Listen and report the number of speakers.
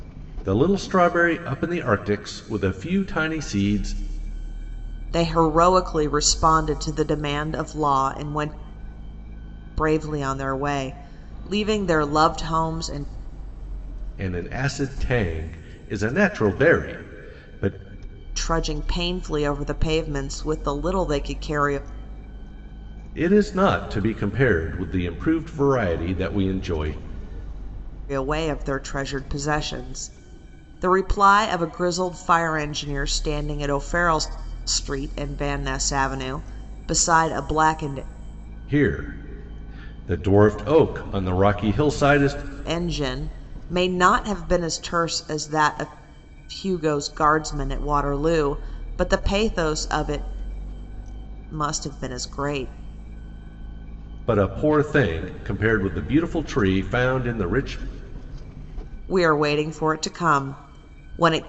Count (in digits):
2